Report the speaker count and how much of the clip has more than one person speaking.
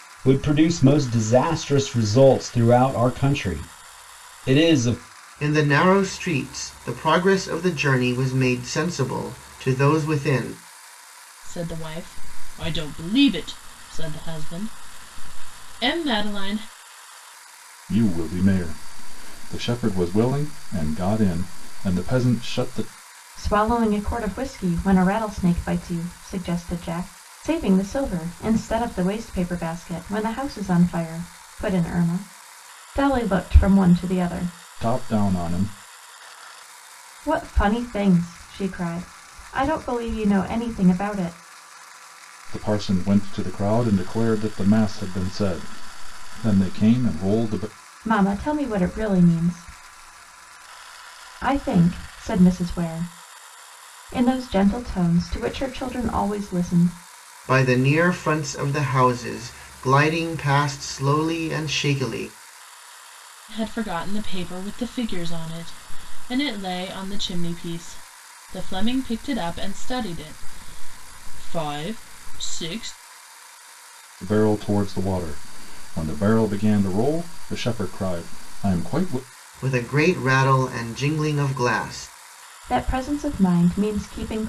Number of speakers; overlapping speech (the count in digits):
5, no overlap